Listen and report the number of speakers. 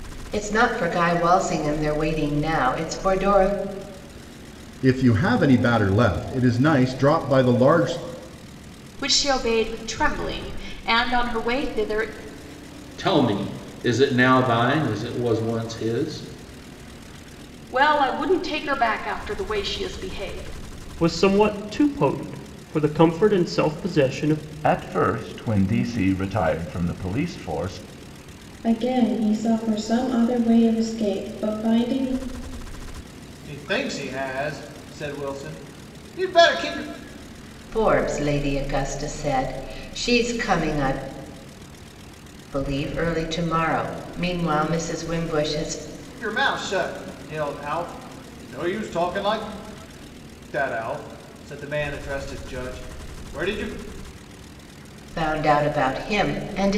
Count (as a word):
nine